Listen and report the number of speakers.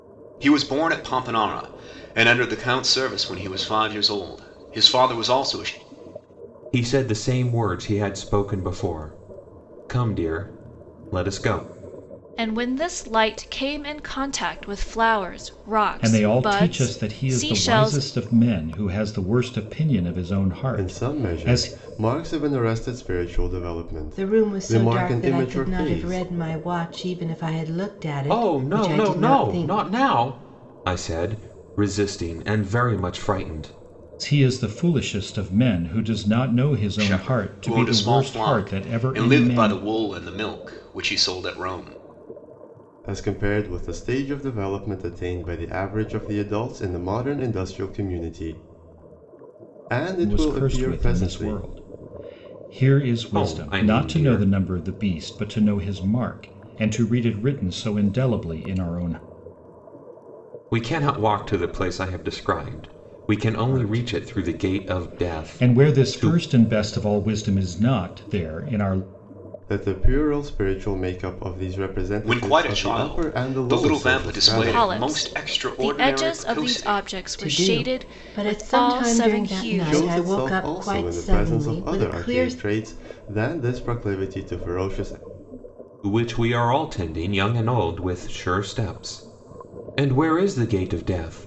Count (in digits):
6